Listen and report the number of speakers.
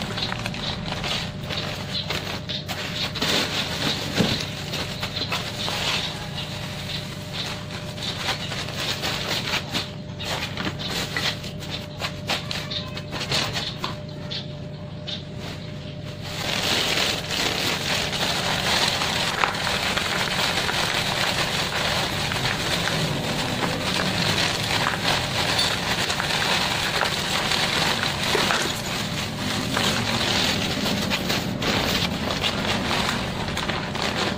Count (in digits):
0